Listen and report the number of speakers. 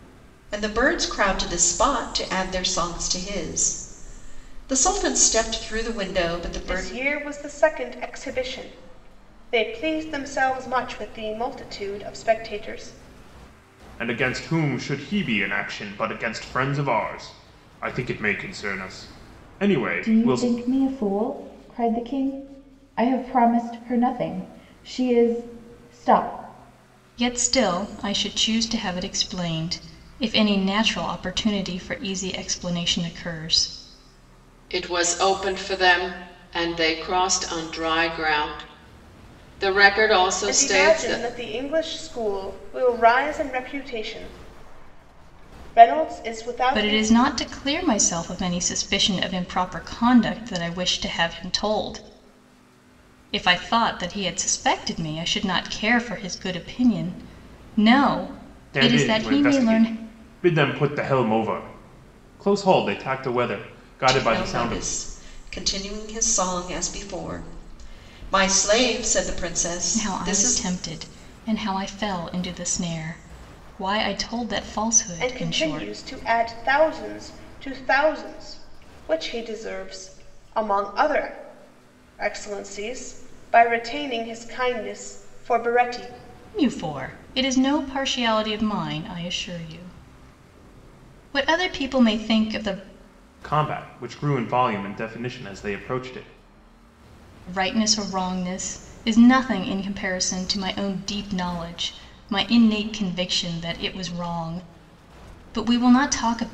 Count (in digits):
6